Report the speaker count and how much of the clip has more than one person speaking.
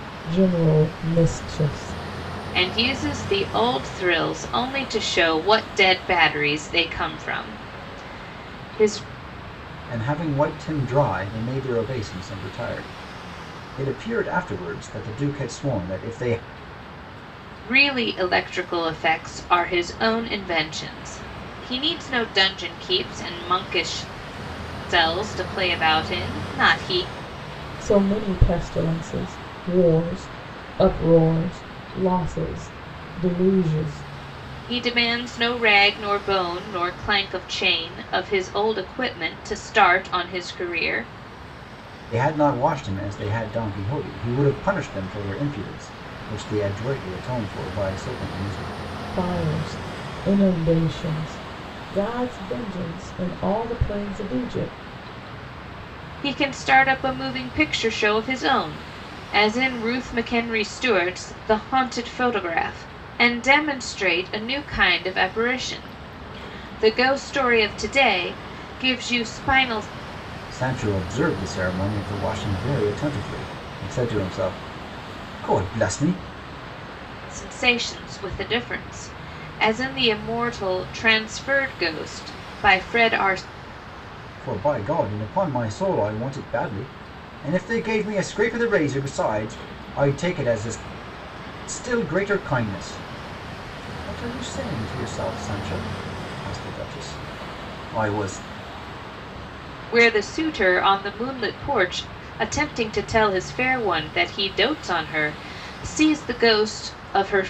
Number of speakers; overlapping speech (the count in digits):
3, no overlap